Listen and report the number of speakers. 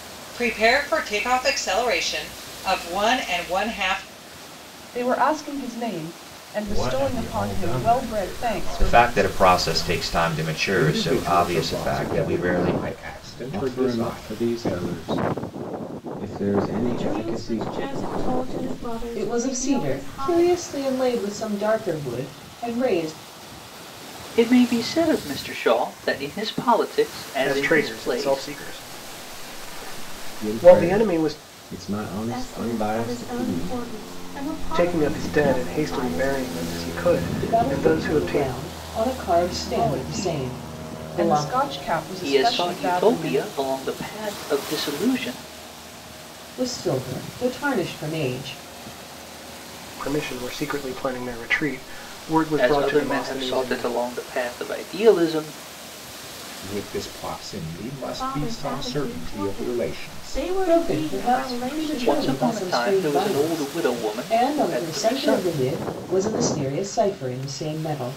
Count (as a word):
ten